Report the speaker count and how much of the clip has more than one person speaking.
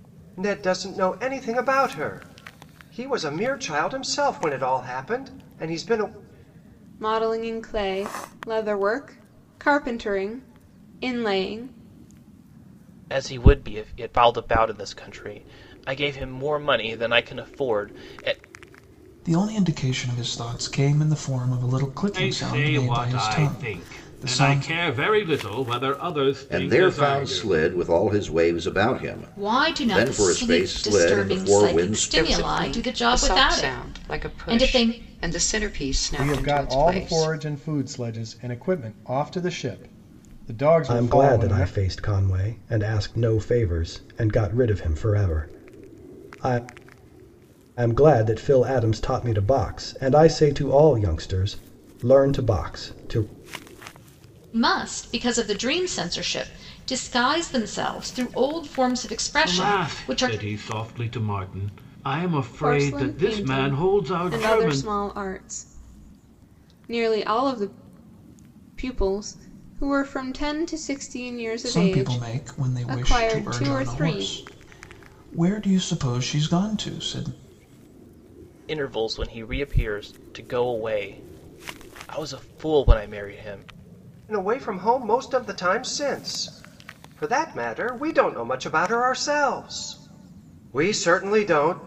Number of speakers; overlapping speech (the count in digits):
10, about 19%